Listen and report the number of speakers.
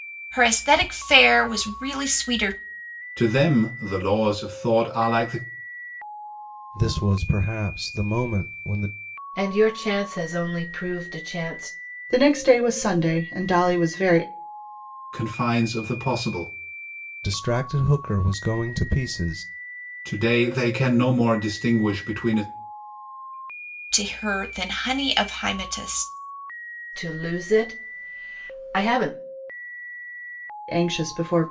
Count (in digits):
5